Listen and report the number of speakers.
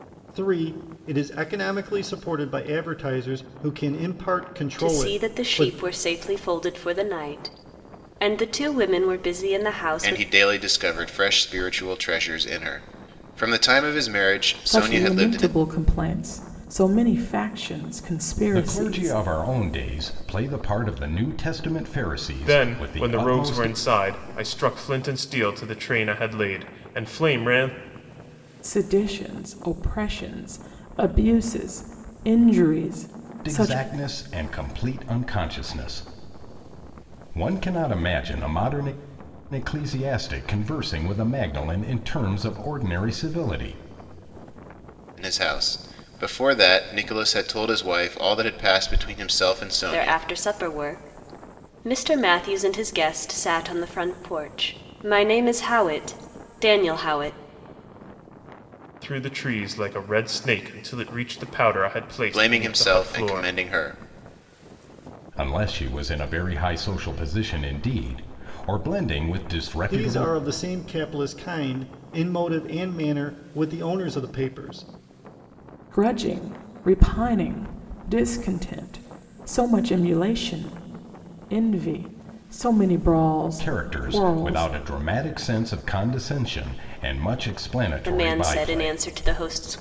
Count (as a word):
six